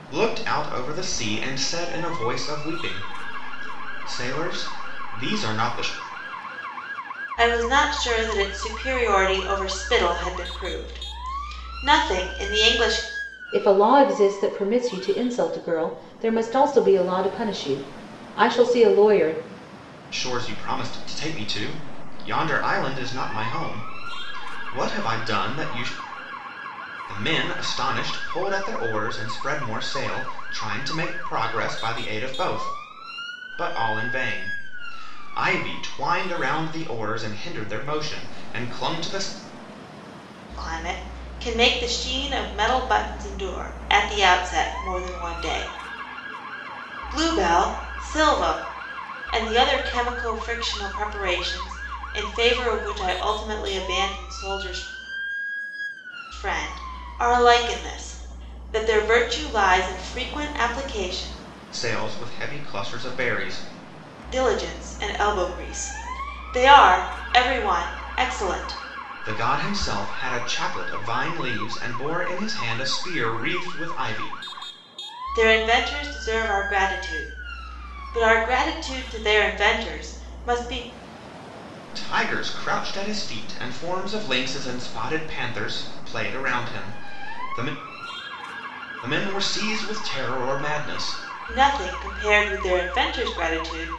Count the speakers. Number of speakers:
3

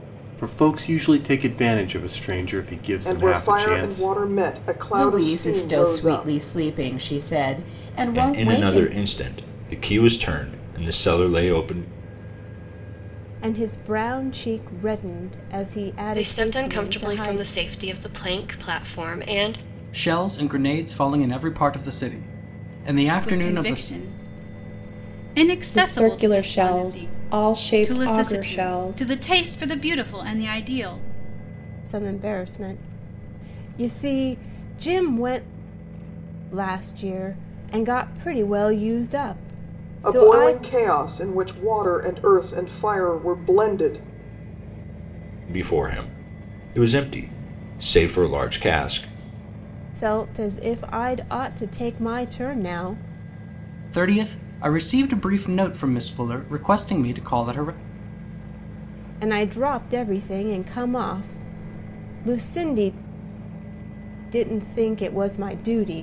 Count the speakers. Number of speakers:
9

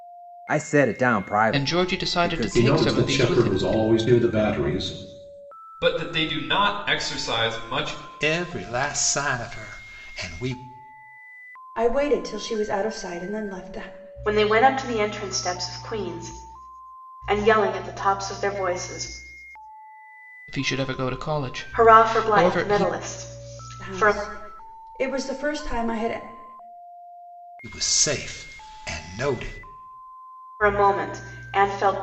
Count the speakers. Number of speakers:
7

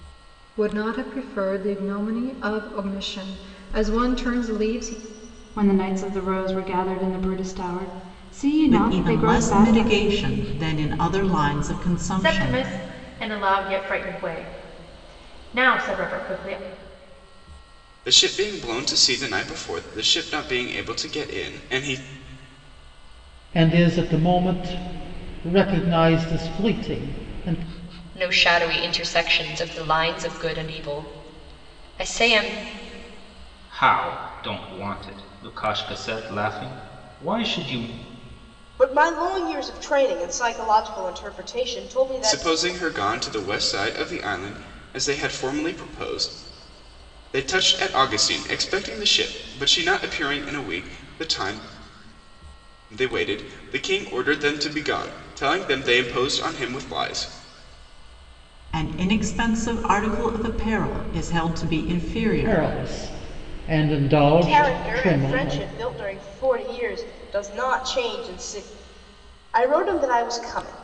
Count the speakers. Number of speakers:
9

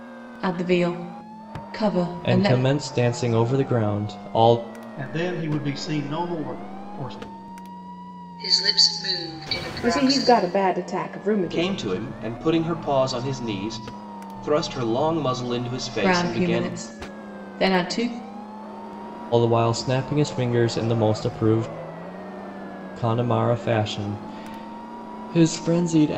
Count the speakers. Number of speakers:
6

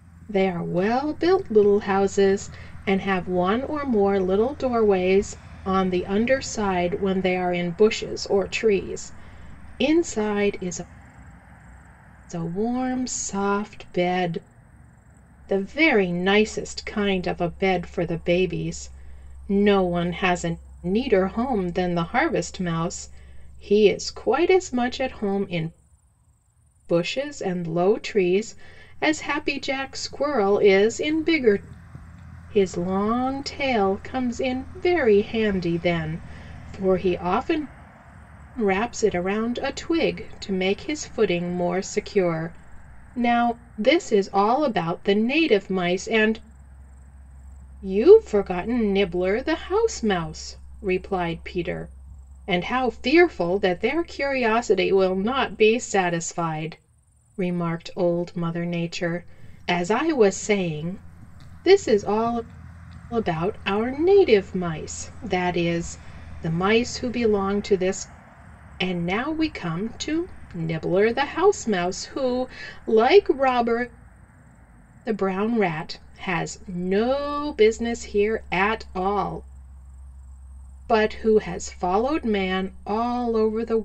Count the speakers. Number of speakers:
1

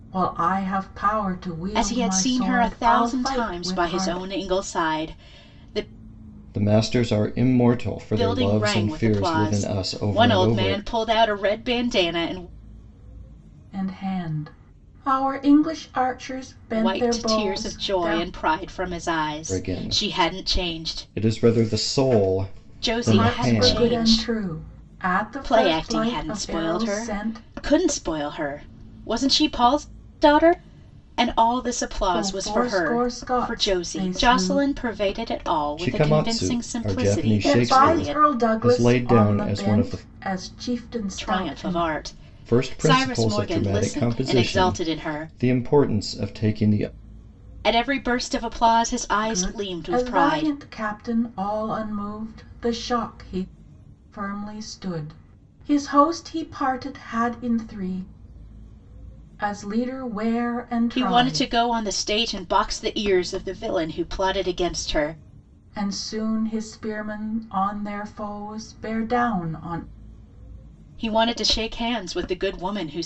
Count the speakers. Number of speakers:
3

